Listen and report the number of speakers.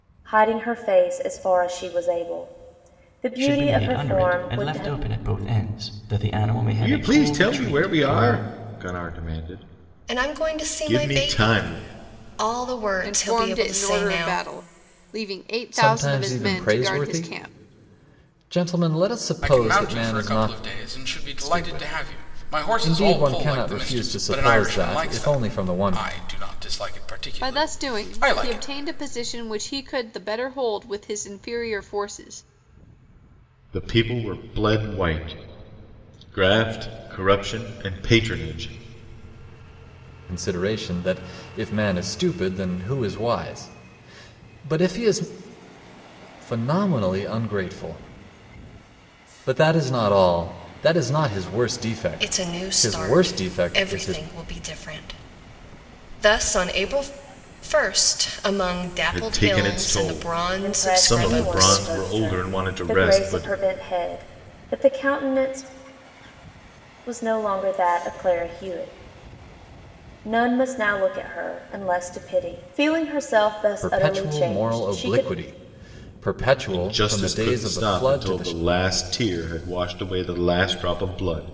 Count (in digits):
7